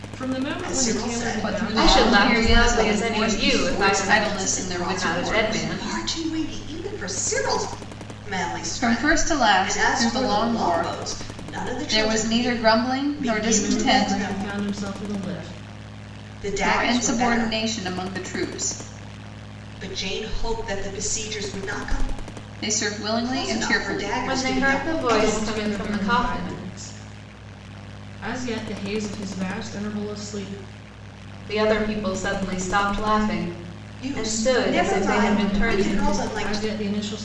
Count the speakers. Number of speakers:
4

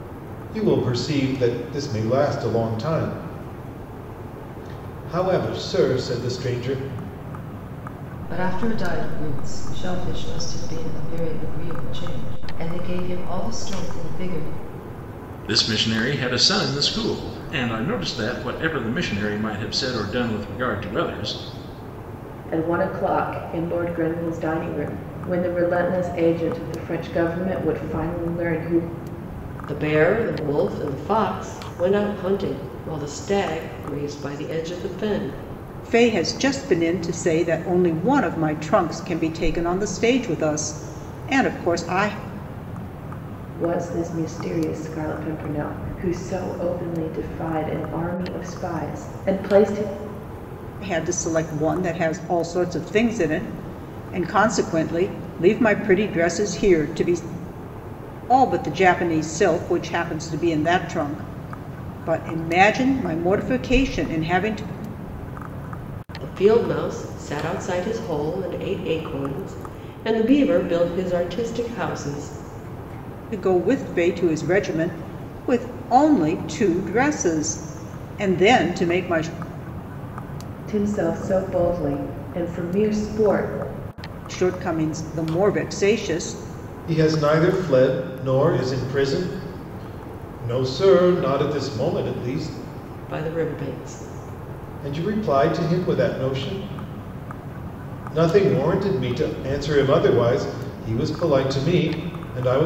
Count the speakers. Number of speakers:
6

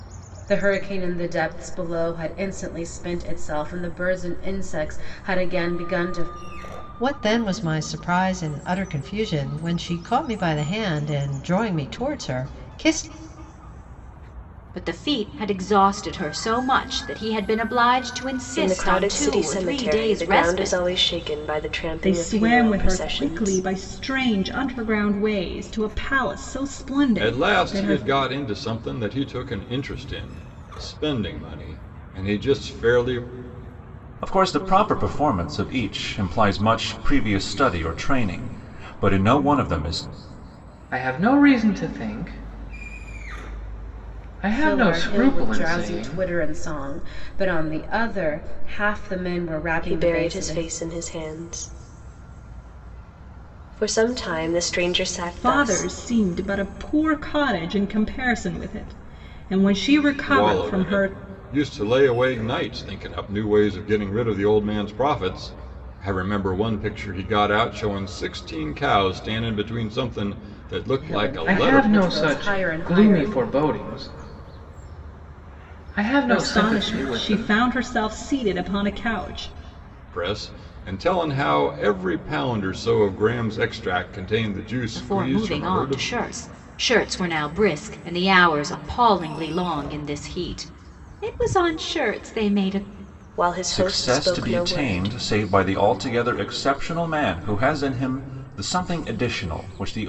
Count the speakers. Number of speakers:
8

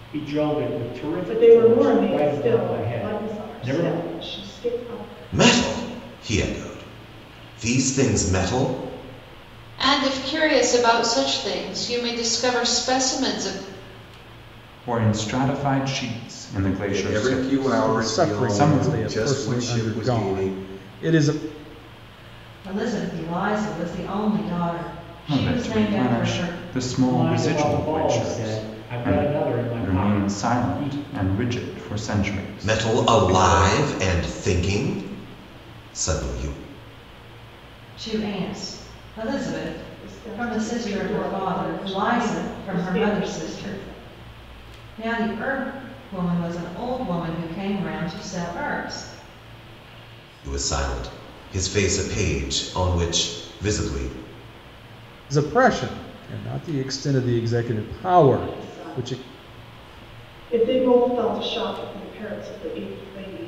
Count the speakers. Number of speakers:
8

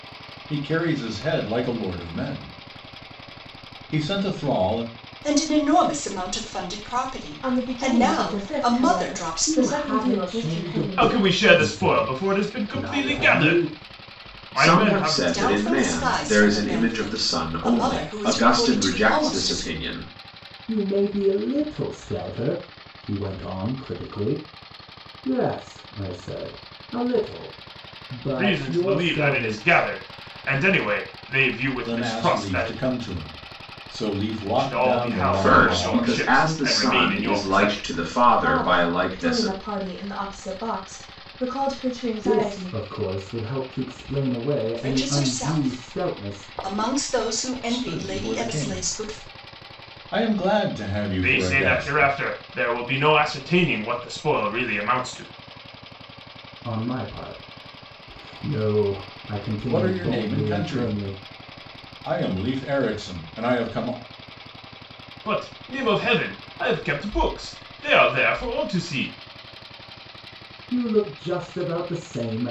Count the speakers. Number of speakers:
6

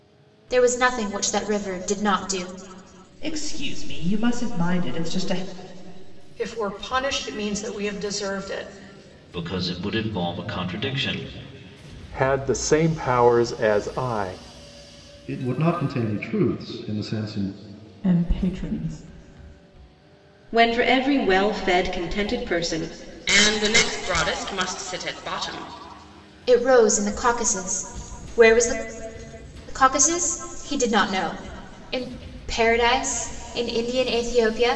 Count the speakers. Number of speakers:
9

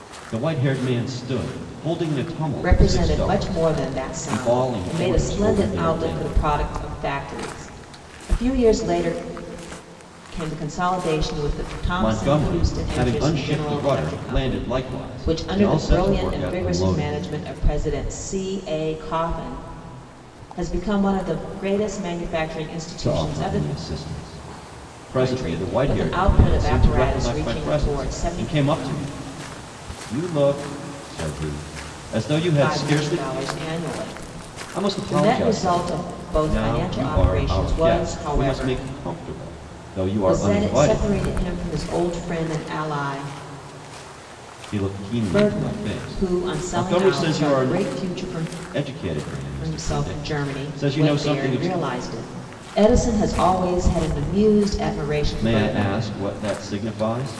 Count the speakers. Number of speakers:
2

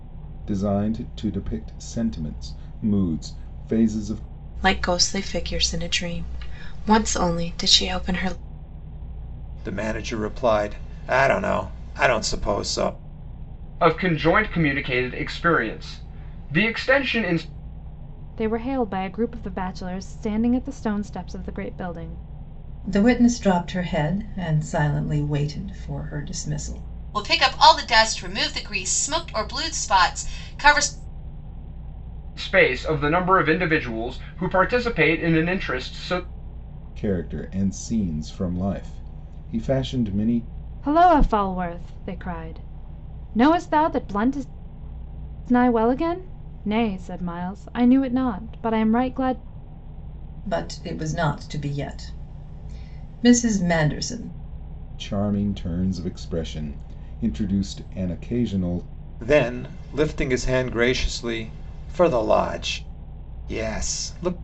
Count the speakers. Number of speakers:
7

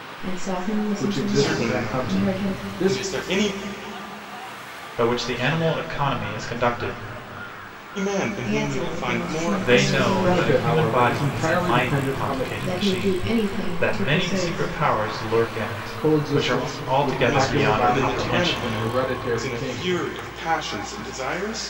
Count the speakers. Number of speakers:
4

